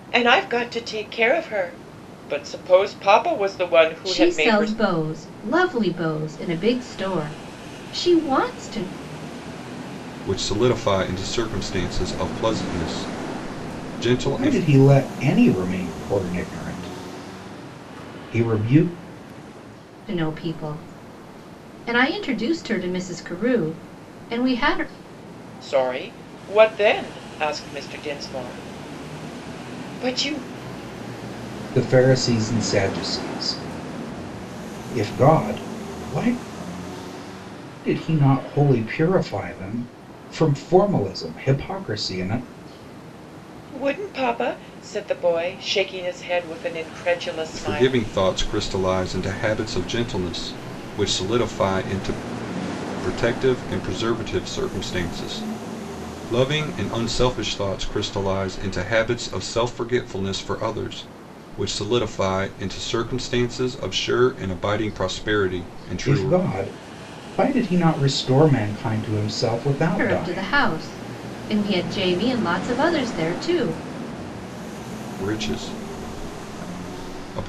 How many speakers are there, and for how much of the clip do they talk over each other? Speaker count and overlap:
four, about 3%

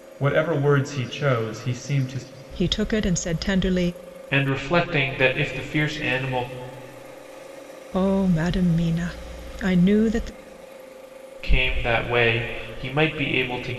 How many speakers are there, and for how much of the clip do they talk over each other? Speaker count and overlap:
three, no overlap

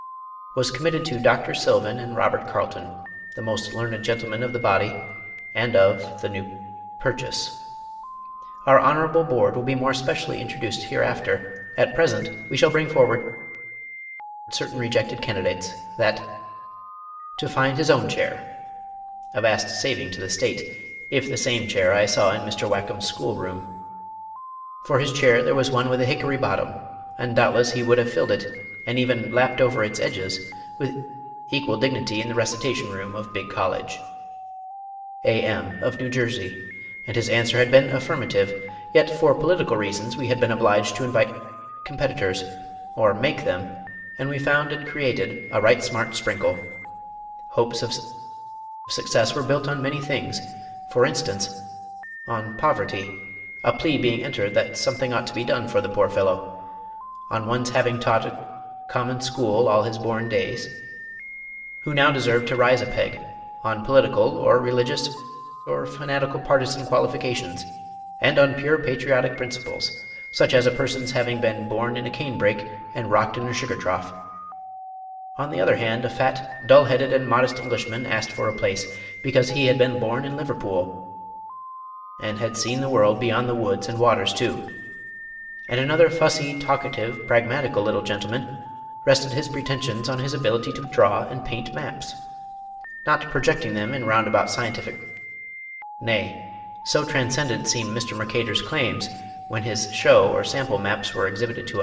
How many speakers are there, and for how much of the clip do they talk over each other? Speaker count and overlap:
one, no overlap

